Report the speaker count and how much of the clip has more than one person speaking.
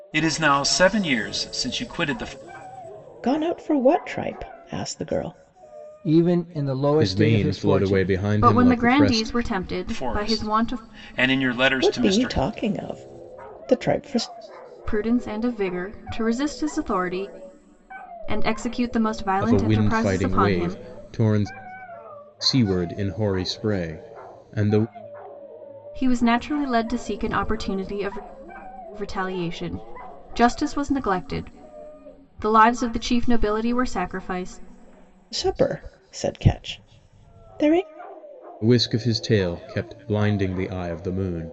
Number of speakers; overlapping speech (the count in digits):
5, about 13%